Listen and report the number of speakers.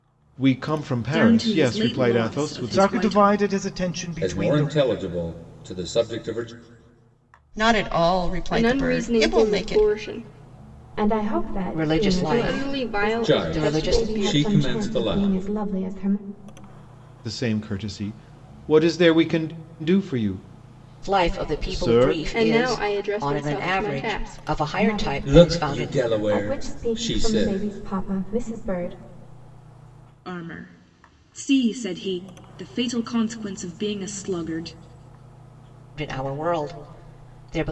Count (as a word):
eight